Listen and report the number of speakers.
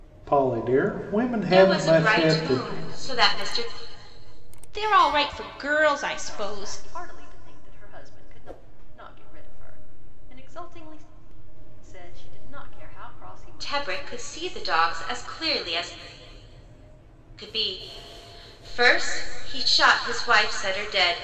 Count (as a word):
four